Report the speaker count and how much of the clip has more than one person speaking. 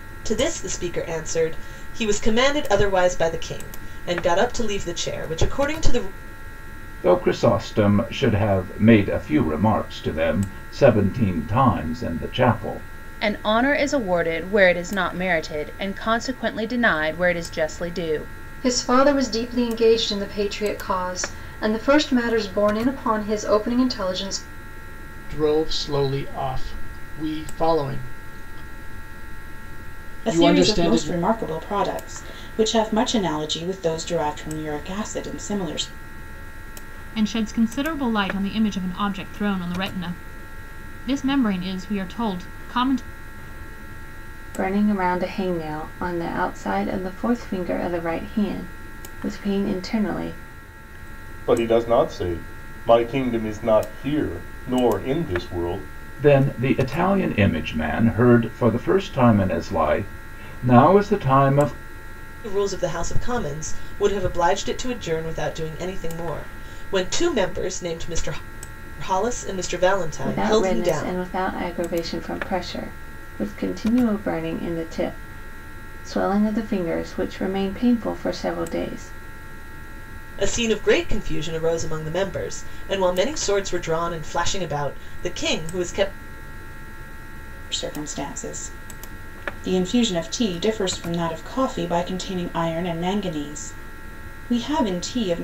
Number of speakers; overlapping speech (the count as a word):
nine, about 2%